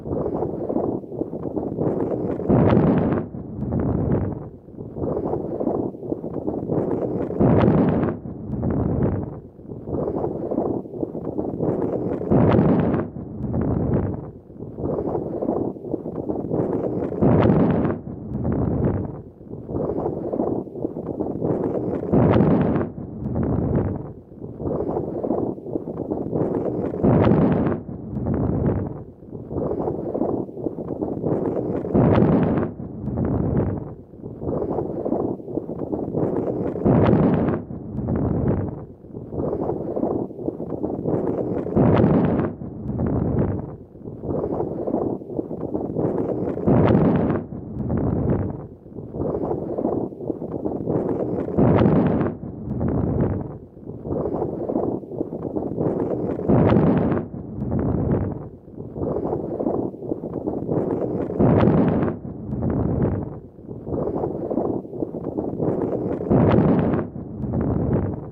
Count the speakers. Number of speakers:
zero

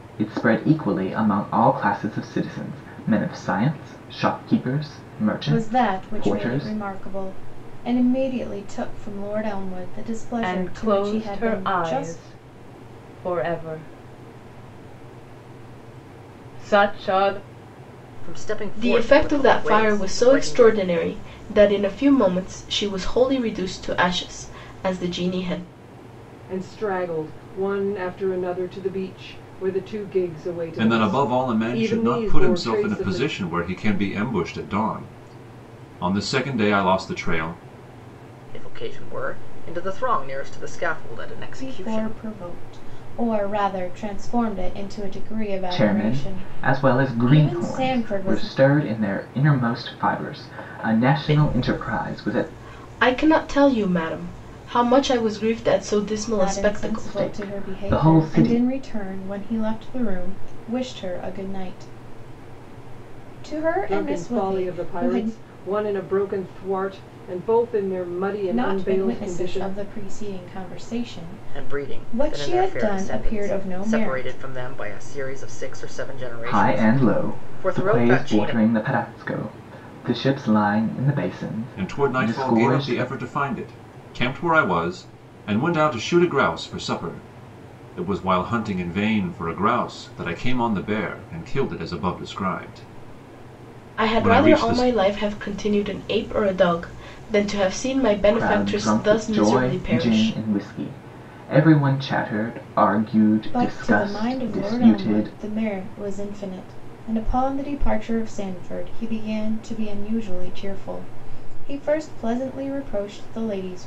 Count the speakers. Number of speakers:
seven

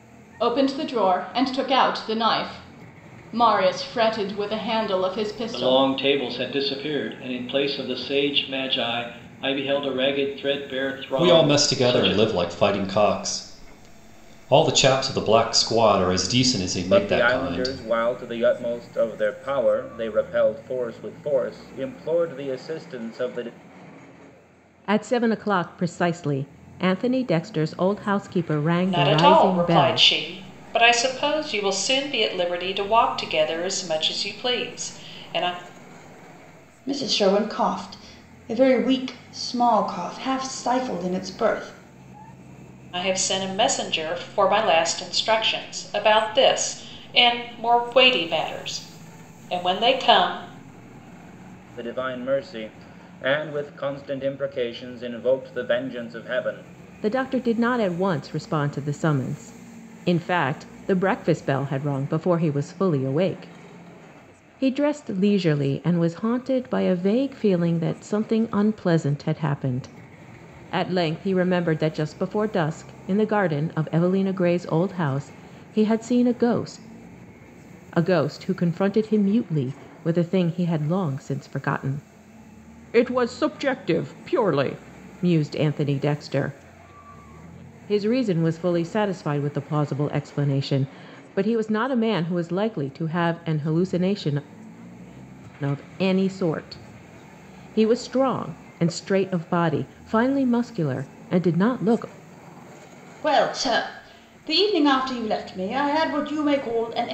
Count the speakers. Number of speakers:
seven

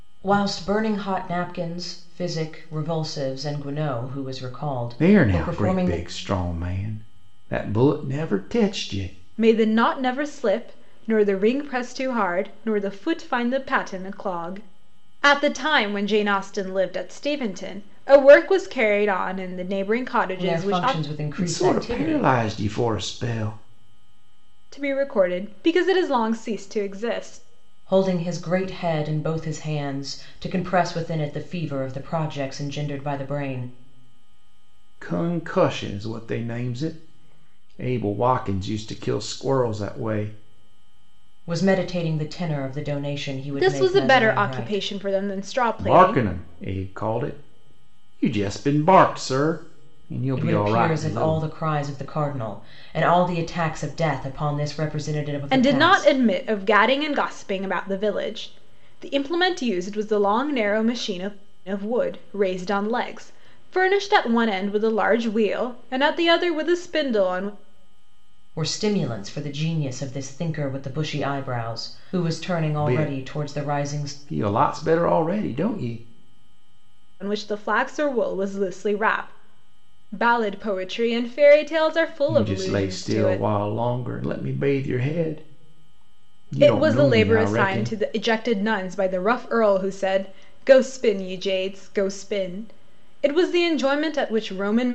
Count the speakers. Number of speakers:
three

